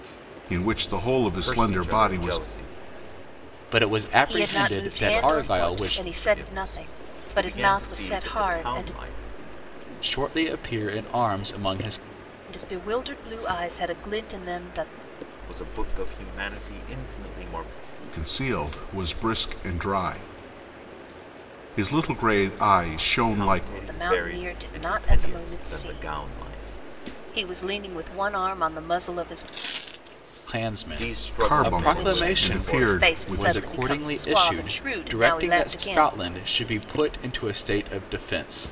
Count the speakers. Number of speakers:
four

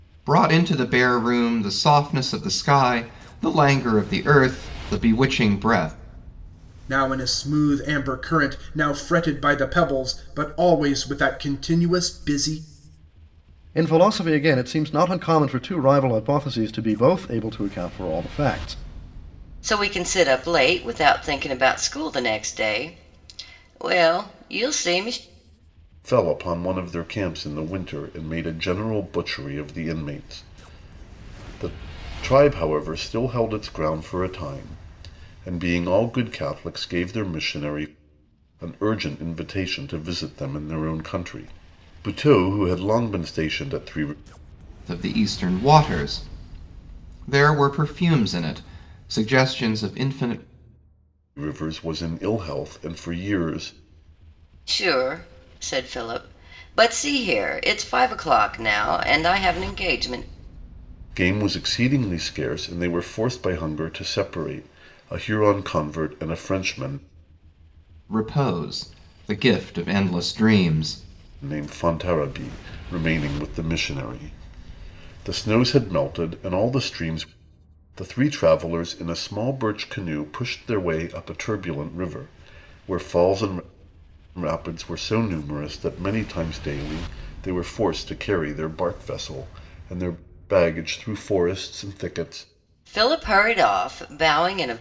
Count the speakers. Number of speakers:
five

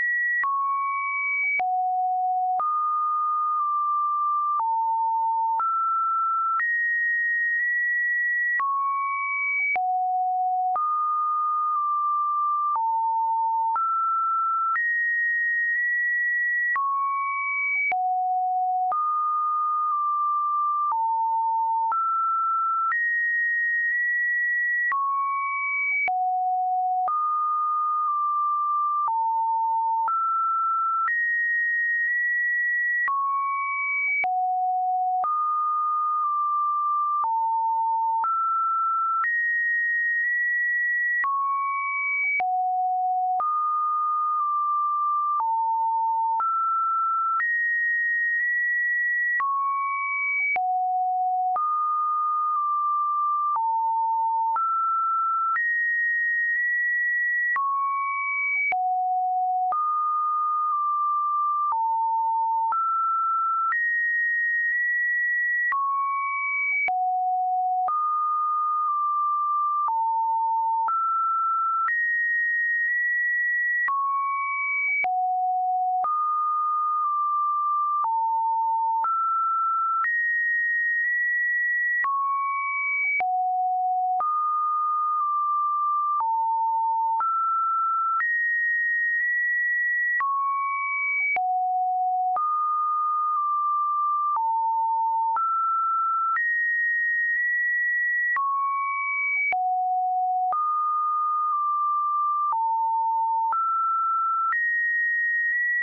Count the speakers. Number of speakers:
zero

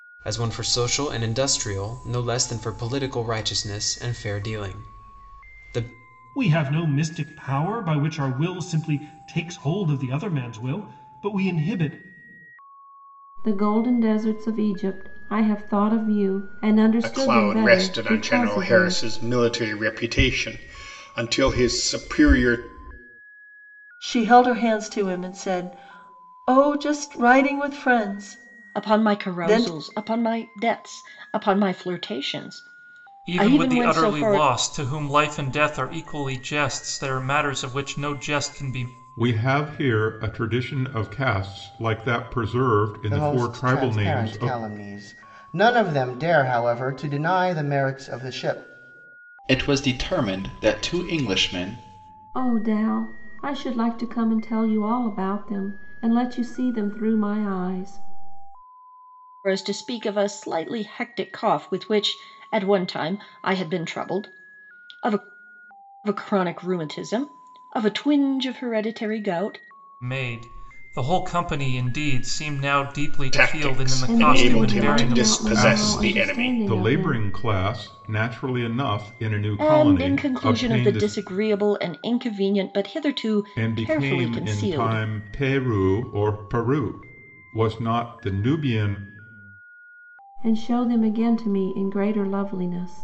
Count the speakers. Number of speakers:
ten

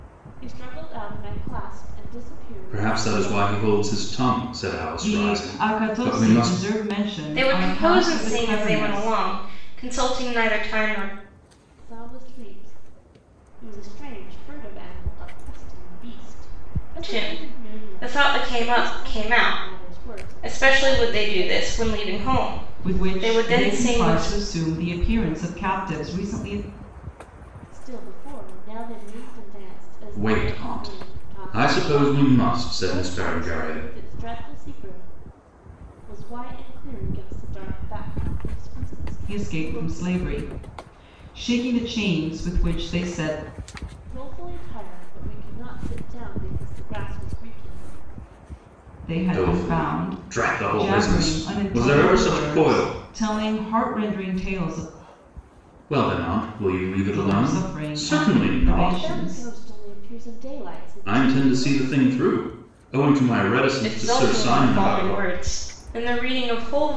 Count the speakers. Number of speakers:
four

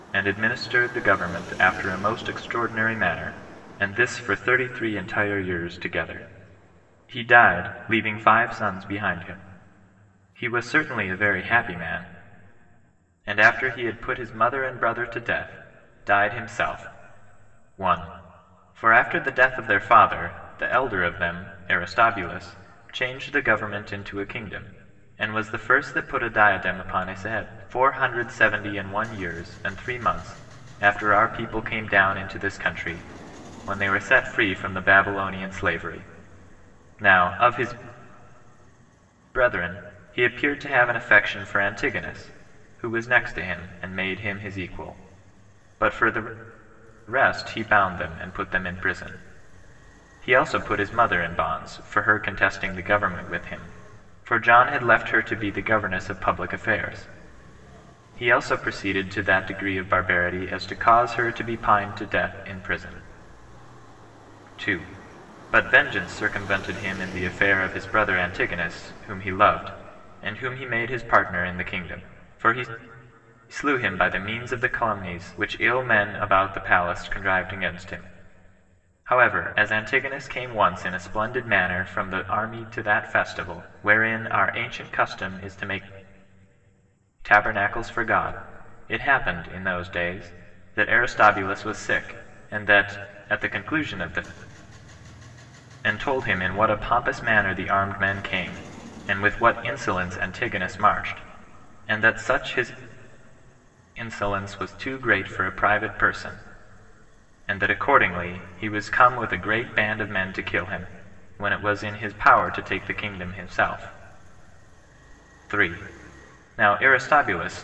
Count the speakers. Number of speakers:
one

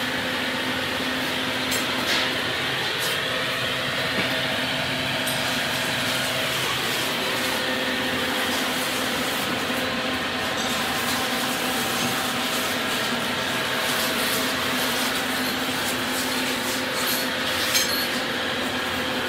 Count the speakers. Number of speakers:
zero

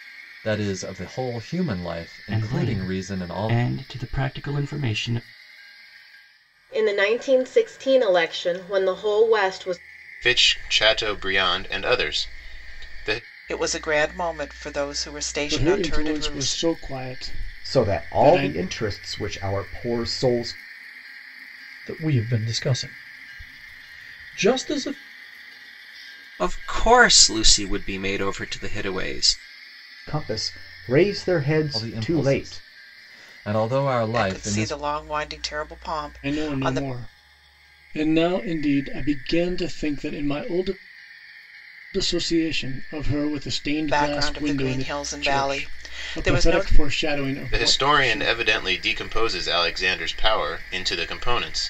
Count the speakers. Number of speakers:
nine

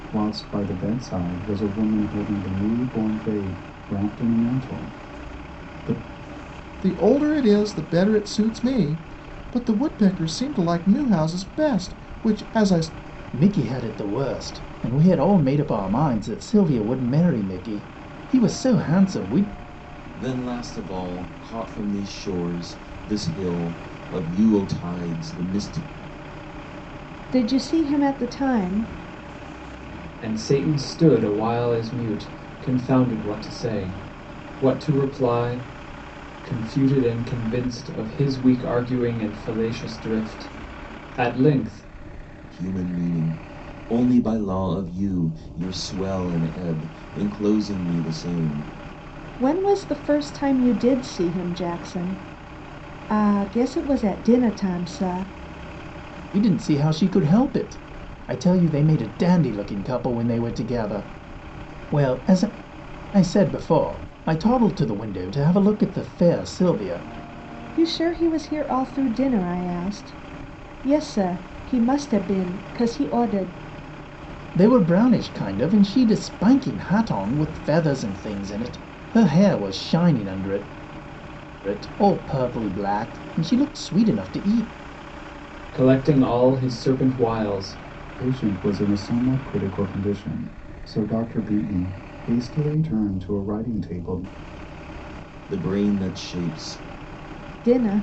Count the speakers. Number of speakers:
six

